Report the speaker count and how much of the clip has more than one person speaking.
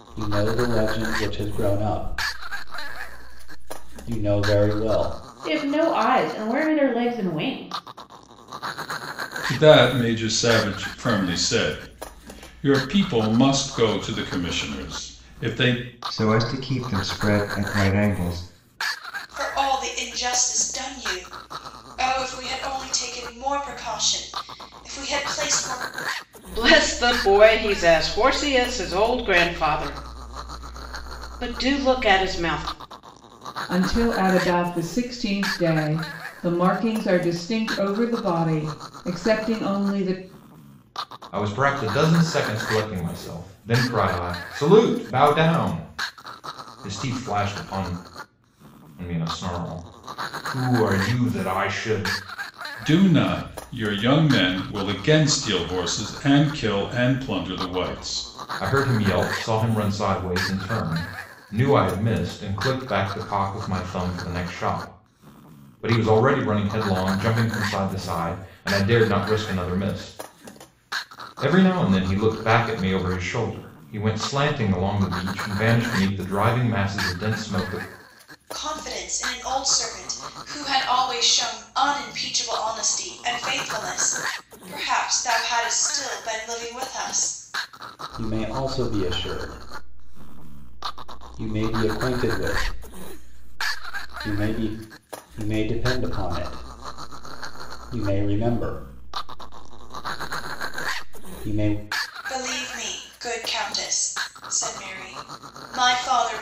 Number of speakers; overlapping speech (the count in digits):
8, no overlap